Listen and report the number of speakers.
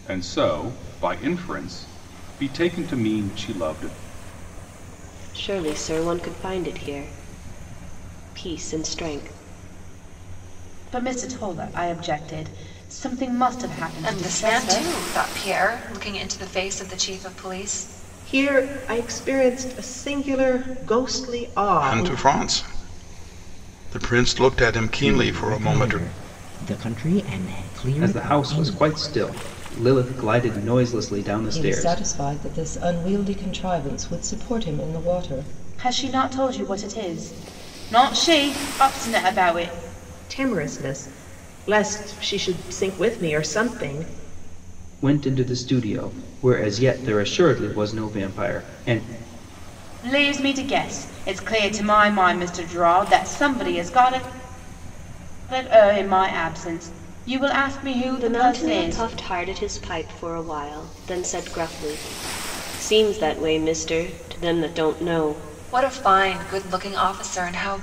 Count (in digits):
9